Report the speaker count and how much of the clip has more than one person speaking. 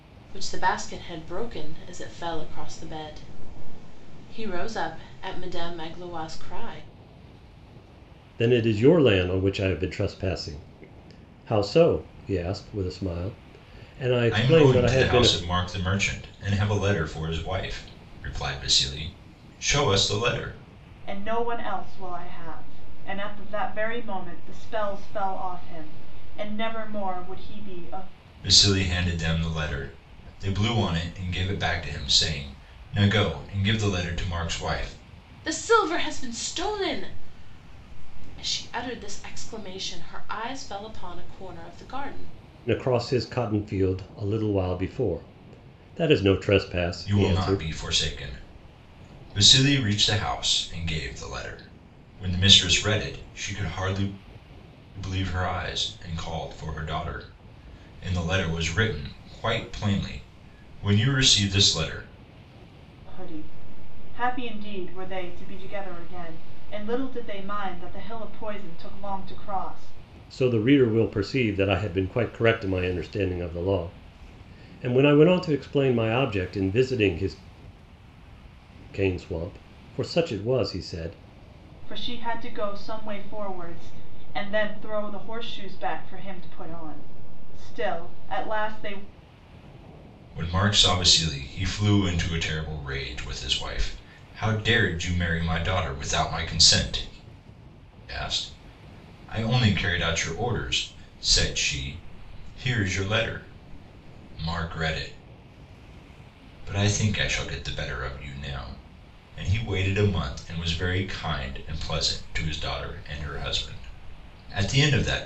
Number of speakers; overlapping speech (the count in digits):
4, about 2%